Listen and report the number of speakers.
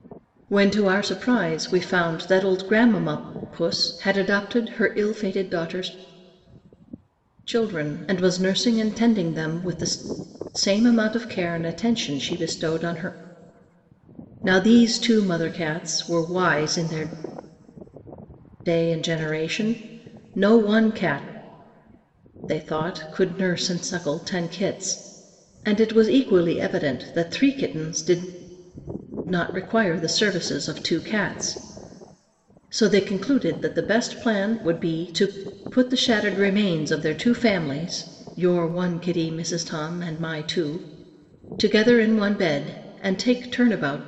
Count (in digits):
1